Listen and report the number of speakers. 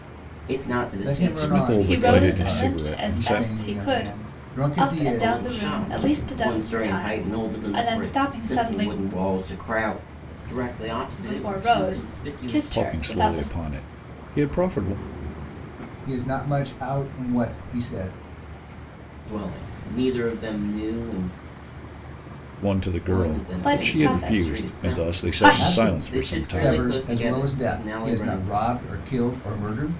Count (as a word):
four